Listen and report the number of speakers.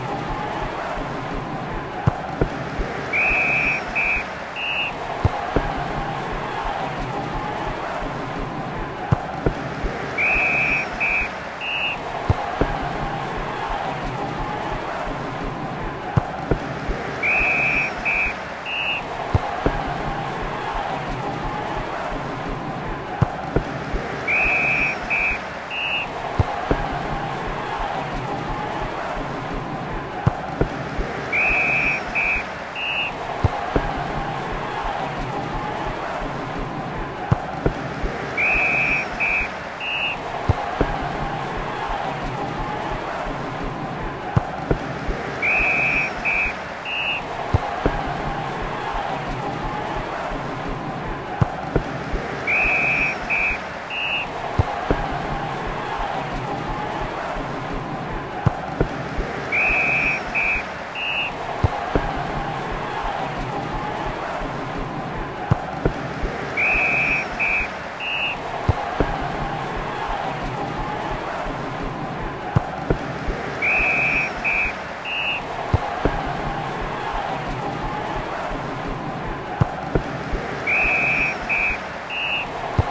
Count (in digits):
0